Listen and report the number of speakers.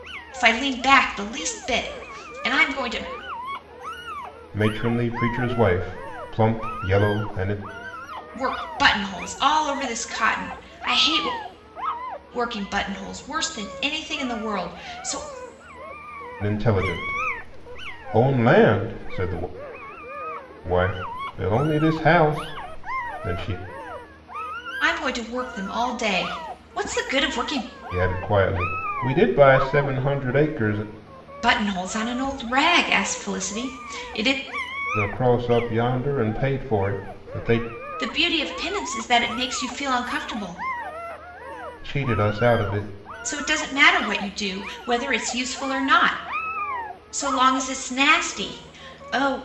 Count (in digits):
2